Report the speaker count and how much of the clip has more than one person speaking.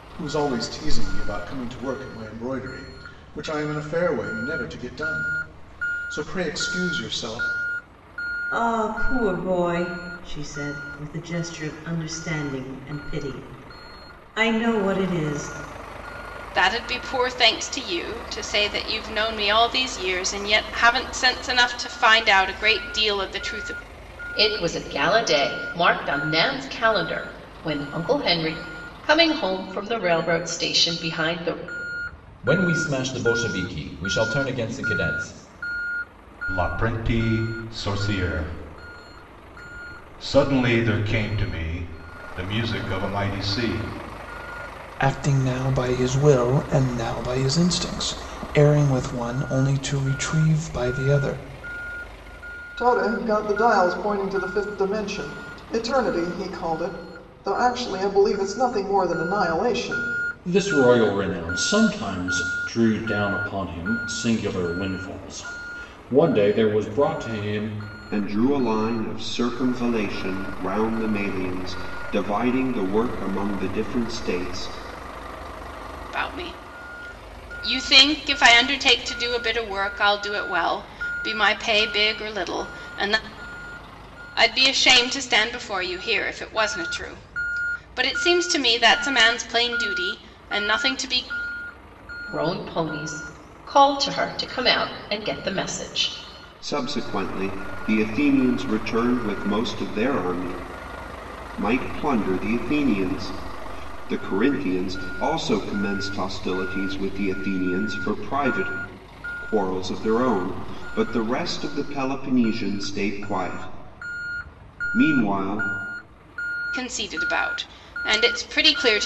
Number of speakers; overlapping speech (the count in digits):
10, no overlap